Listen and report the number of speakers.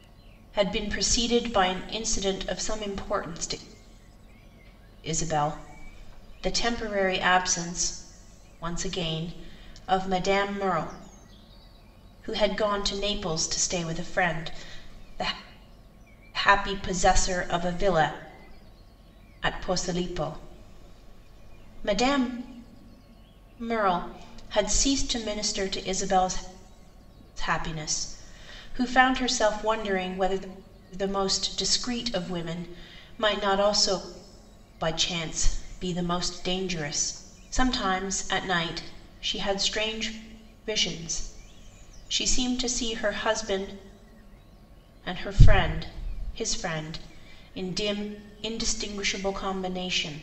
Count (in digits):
1